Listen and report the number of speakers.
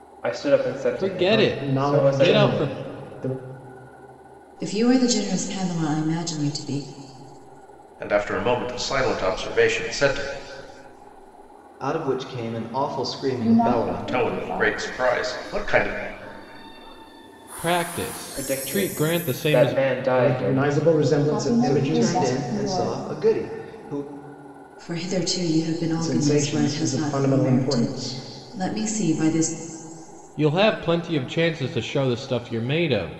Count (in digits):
7